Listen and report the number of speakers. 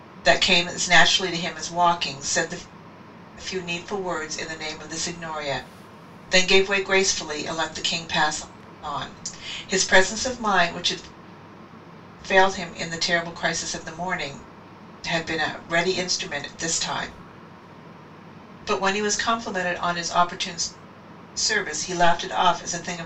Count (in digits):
1